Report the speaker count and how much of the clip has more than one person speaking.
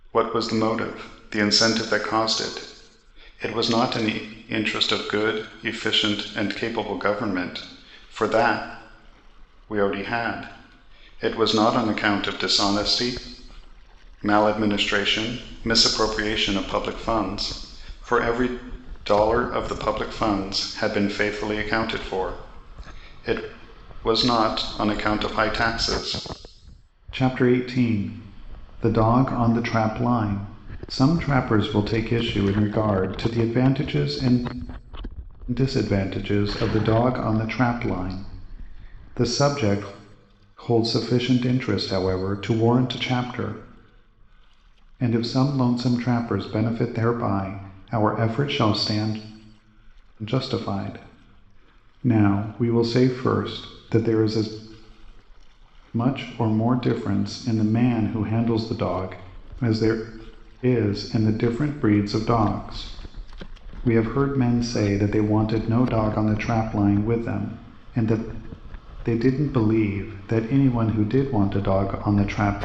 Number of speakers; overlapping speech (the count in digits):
1, no overlap